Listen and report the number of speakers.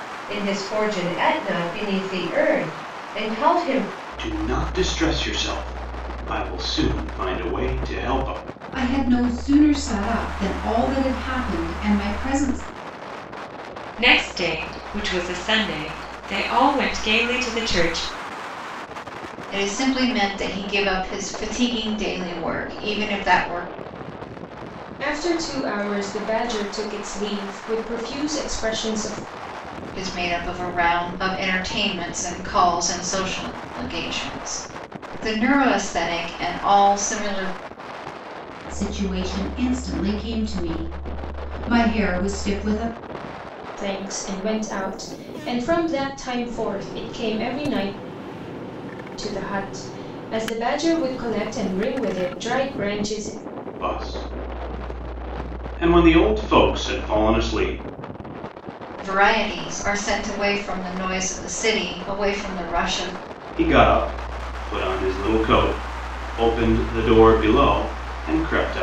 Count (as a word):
six